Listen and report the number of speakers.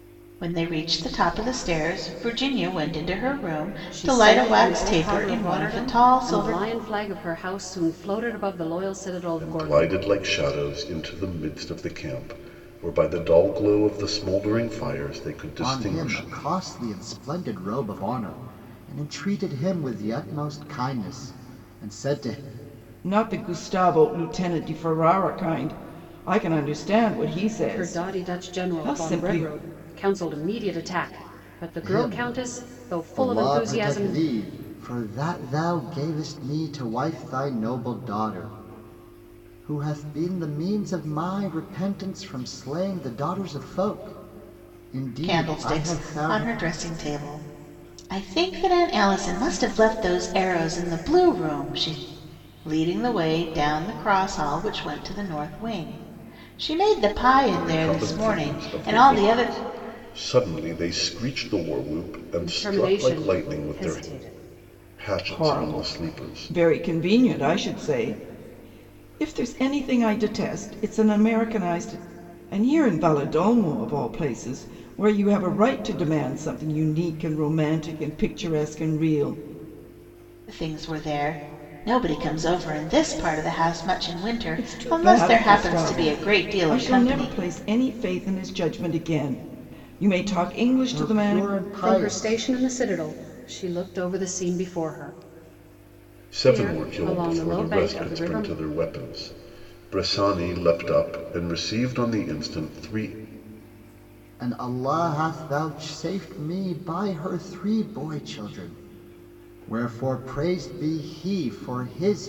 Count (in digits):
5